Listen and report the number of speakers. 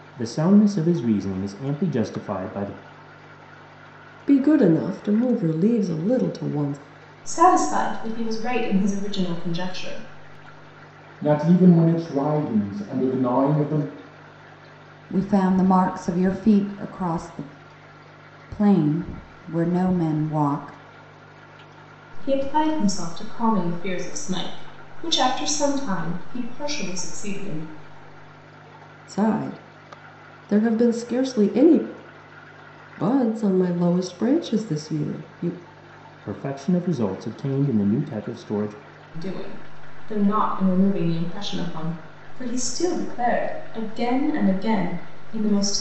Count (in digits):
5